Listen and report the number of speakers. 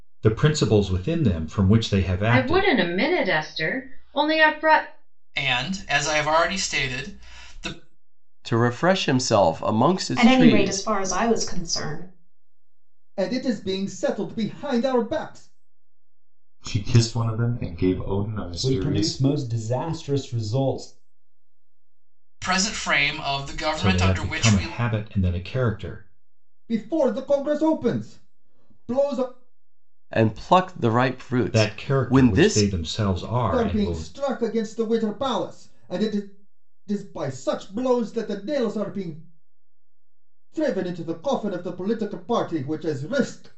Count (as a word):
eight